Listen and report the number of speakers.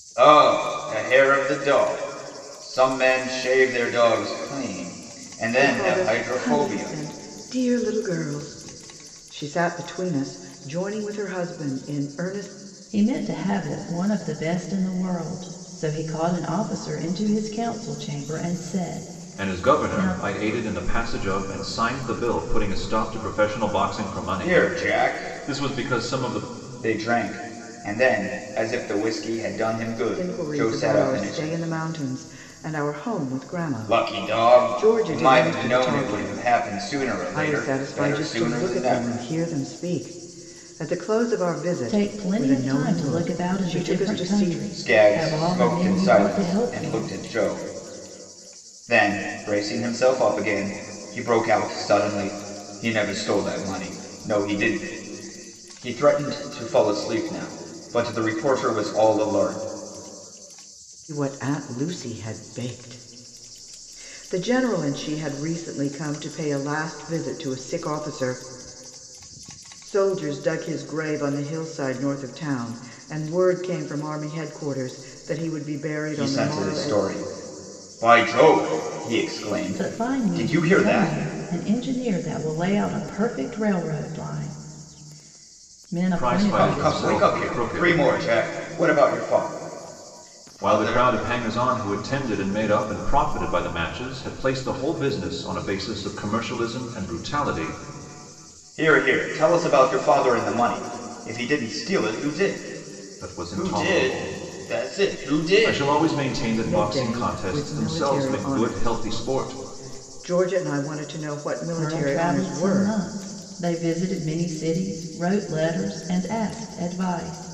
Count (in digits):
4